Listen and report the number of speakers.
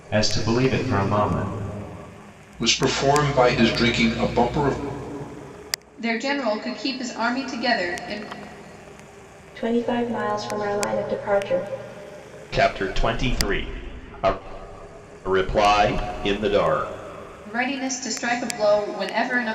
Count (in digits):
5